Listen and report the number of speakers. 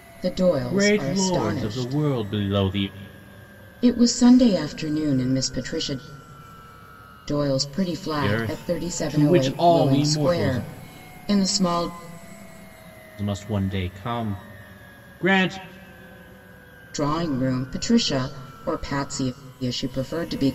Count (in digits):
2